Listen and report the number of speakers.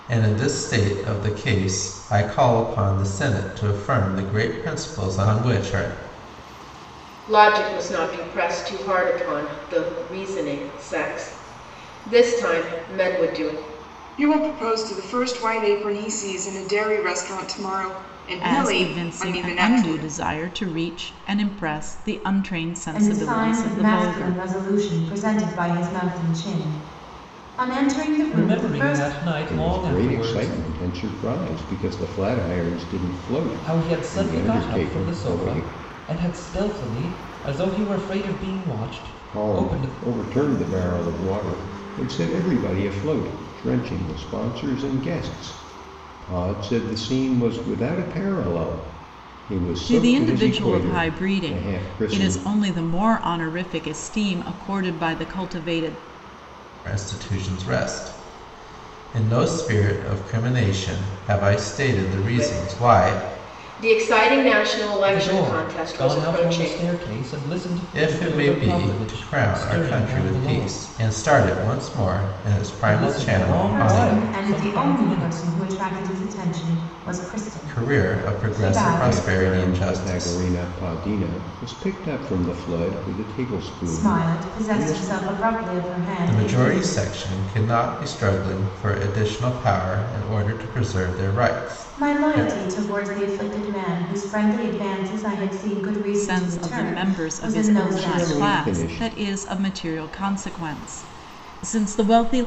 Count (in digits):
7